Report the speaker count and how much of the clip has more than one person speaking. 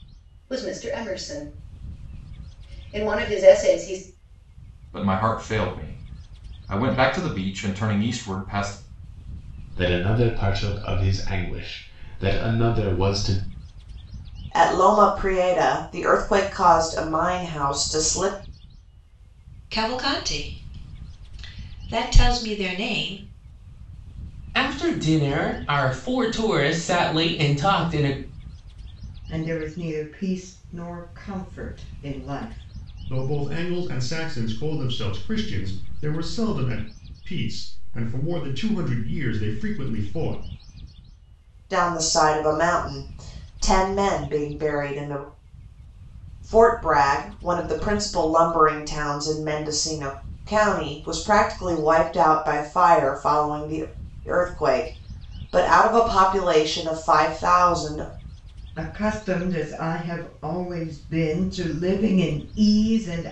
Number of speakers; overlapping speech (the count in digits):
8, no overlap